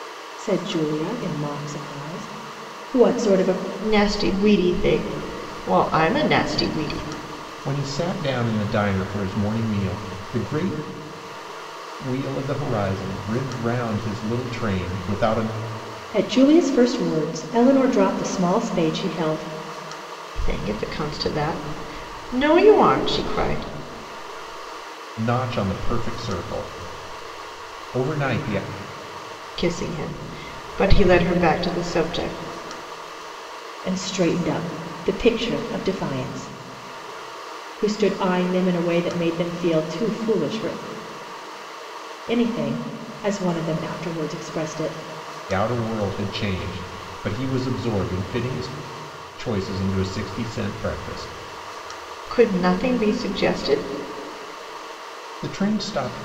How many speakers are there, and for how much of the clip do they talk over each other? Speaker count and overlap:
3, no overlap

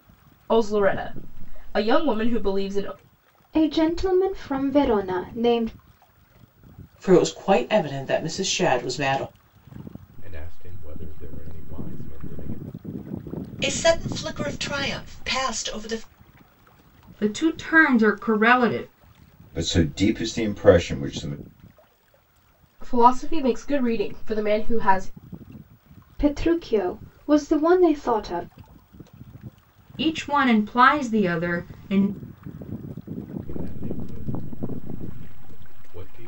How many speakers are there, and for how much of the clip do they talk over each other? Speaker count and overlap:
7, no overlap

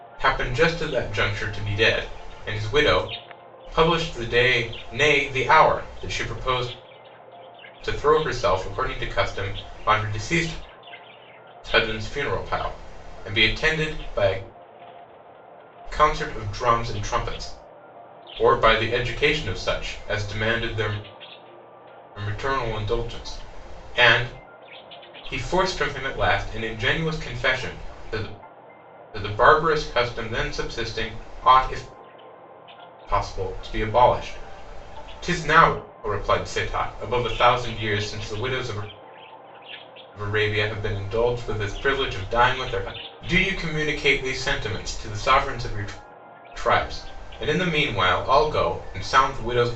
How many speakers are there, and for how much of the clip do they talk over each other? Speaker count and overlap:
1, no overlap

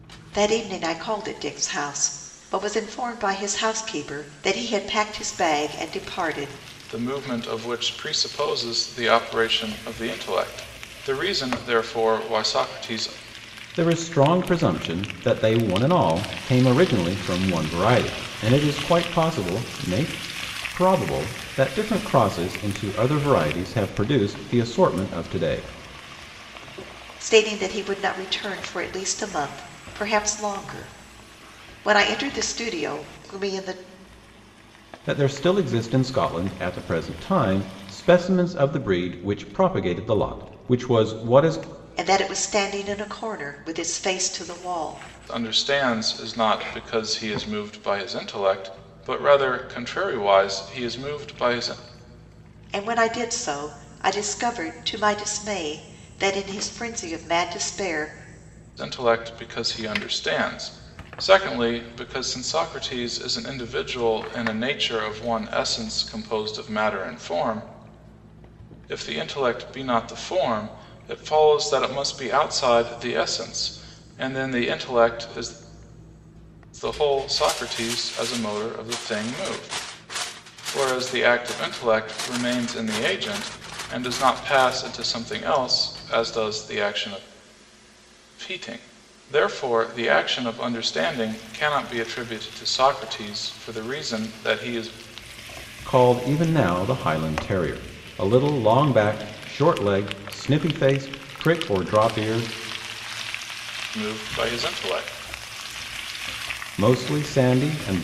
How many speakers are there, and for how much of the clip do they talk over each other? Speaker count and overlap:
3, no overlap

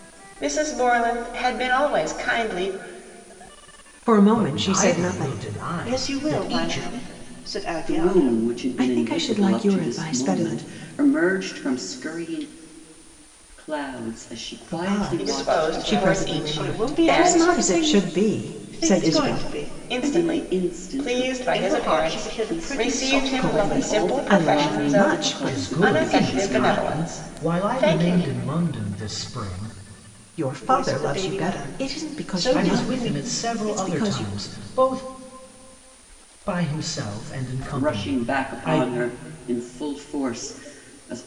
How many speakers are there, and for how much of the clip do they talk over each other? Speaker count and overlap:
5, about 53%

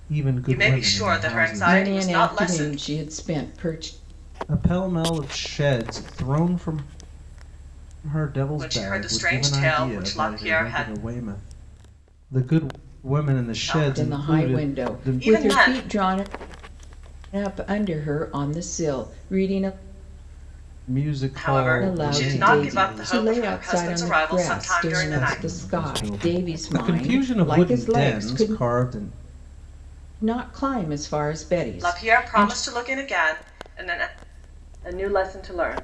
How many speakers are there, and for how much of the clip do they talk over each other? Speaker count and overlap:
3, about 42%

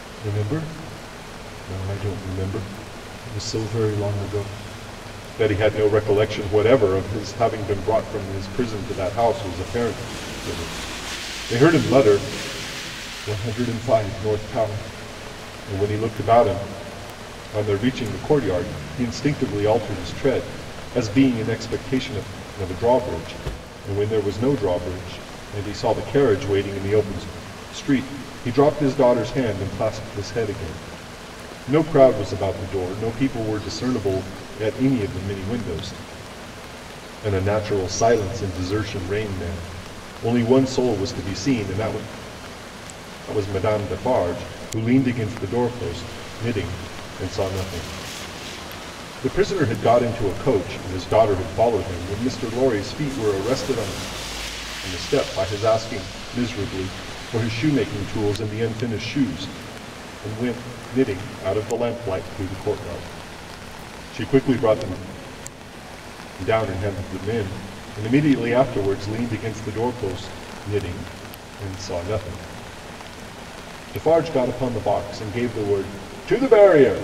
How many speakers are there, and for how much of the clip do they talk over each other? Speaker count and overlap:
1, no overlap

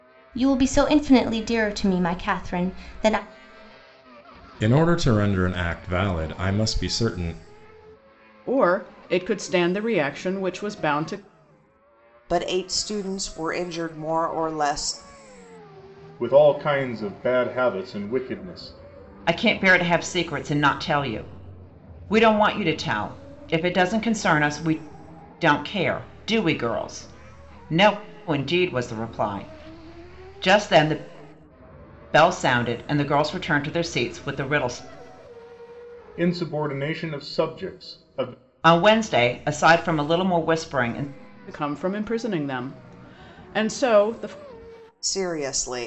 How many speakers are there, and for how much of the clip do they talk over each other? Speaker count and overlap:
6, no overlap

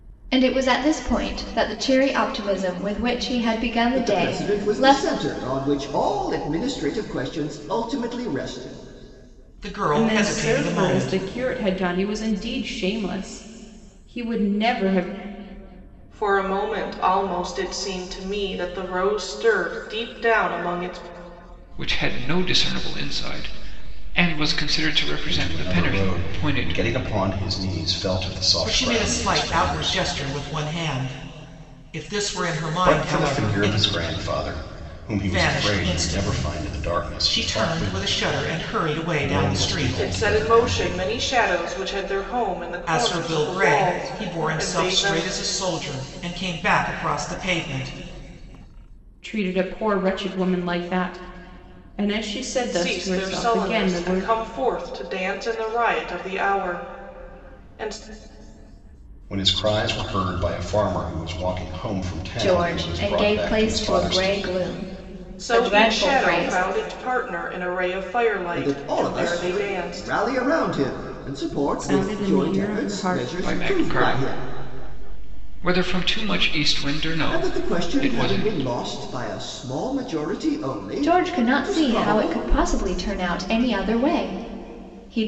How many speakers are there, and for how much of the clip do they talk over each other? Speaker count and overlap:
7, about 30%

